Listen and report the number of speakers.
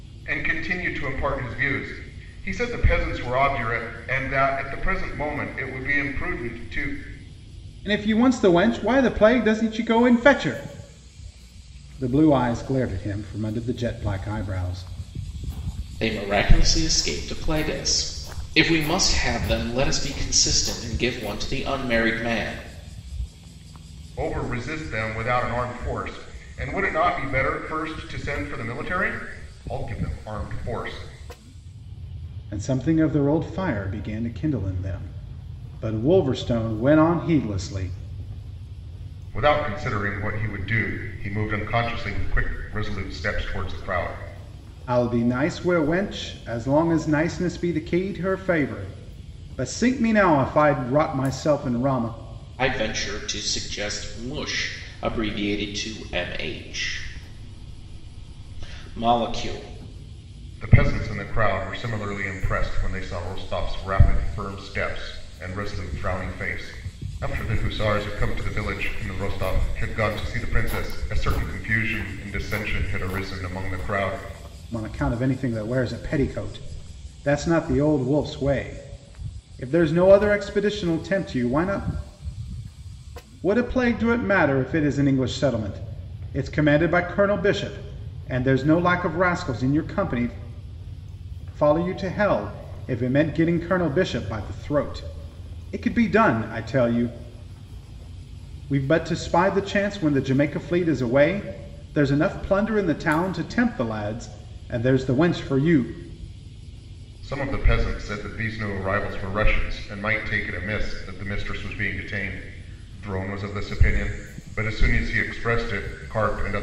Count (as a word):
three